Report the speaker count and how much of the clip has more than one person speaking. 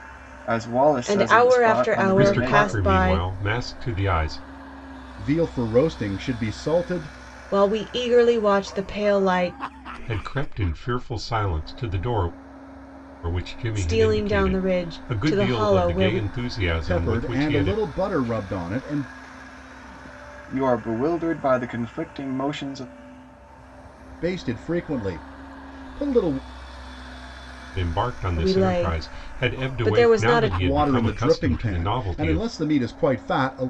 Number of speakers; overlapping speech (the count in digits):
4, about 29%